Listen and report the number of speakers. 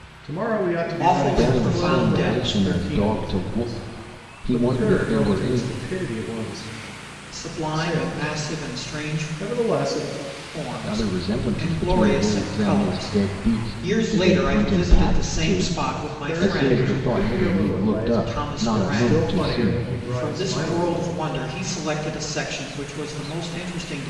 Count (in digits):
3